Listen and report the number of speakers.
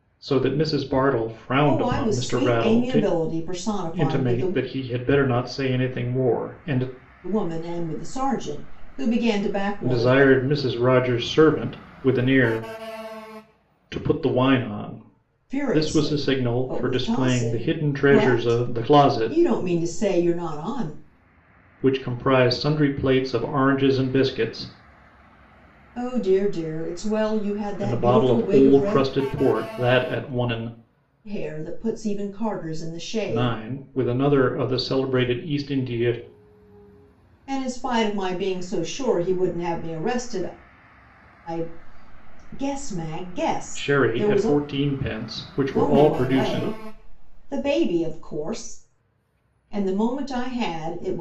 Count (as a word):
two